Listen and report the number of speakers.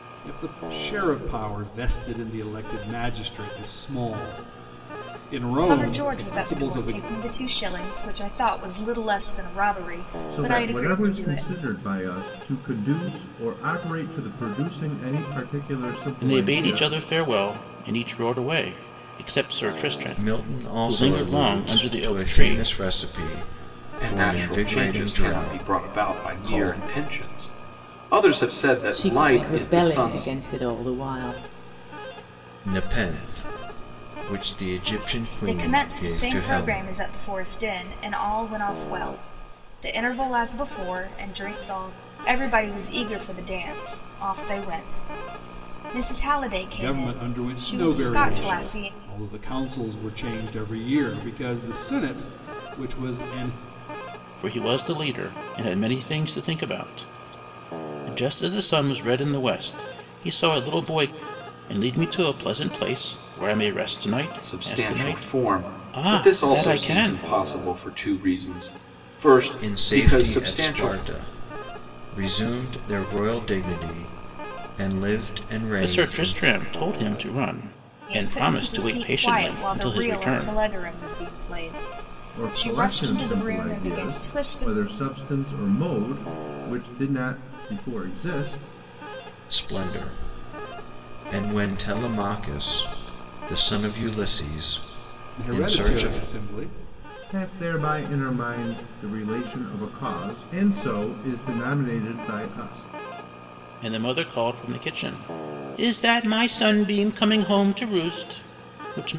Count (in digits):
7